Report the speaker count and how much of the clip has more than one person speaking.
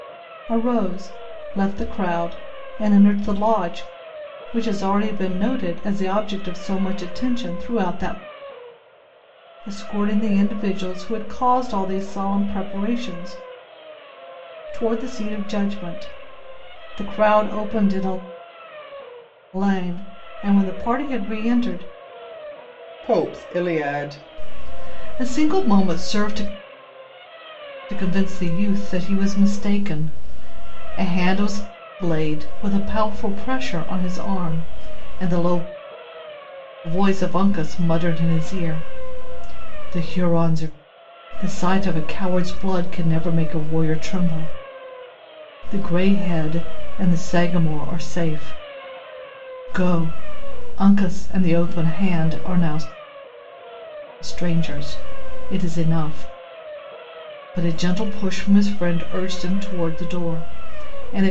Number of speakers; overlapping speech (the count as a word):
one, no overlap